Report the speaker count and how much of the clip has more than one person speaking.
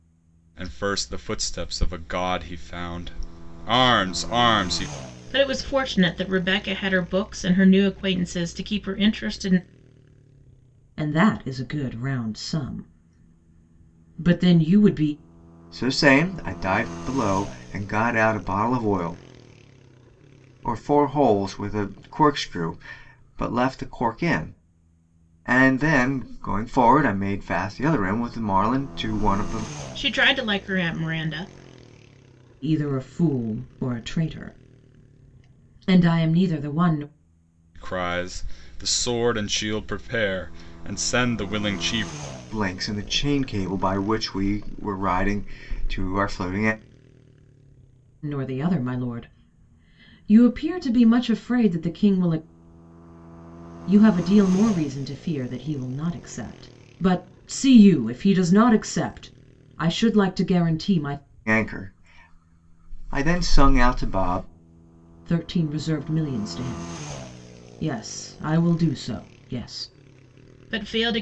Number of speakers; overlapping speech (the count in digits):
4, no overlap